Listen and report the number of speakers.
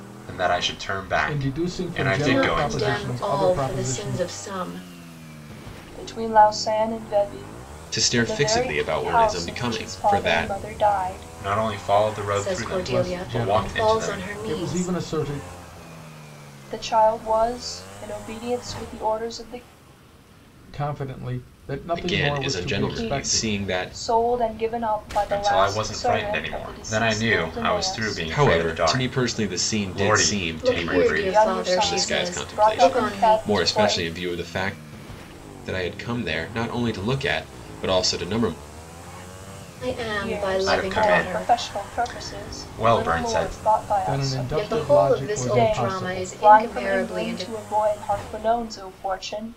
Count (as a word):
five